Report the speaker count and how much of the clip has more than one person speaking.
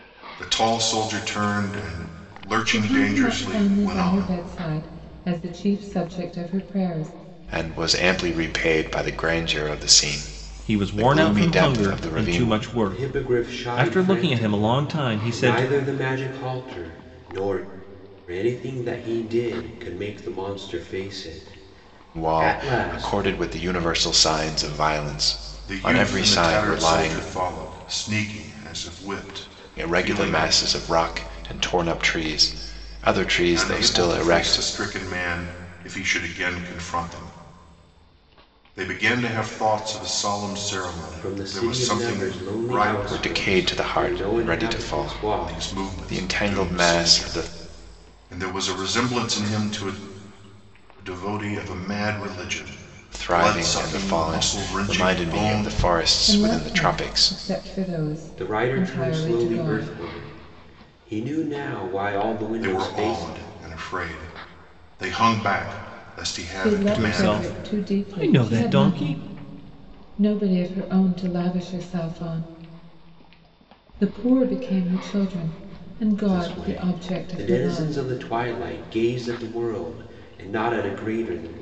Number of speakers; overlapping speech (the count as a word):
five, about 35%